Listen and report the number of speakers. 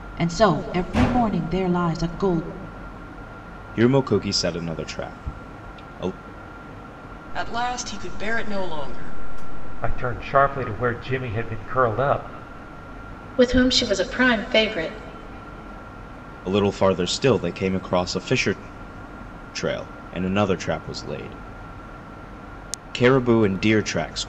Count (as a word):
five